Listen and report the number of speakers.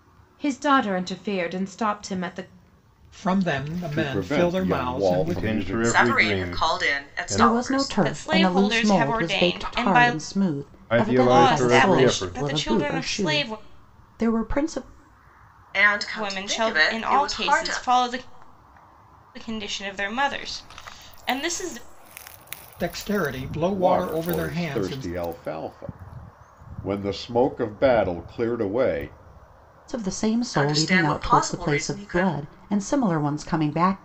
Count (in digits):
7